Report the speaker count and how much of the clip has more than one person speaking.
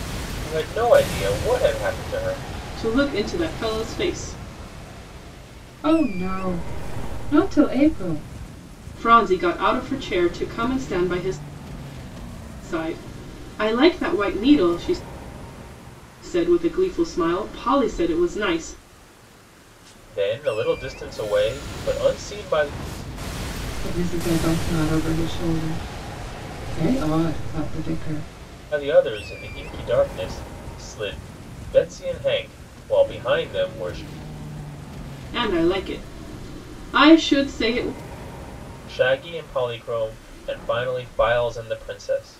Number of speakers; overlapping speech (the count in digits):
3, no overlap